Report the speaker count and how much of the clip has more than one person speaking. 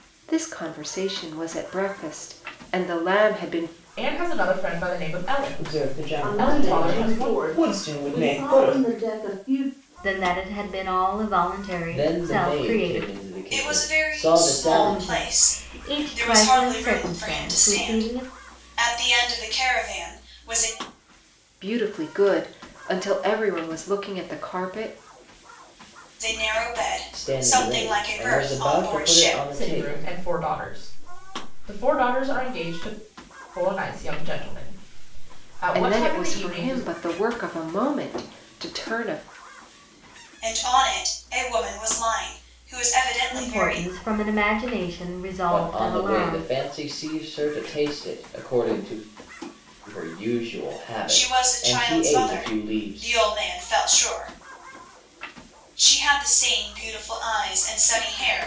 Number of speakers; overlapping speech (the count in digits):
7, about 29%